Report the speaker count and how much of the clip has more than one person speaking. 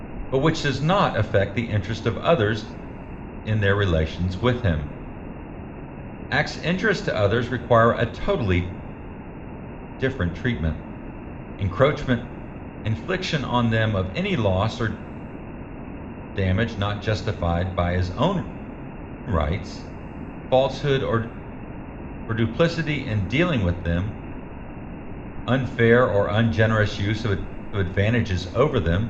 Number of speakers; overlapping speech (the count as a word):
one, no overlap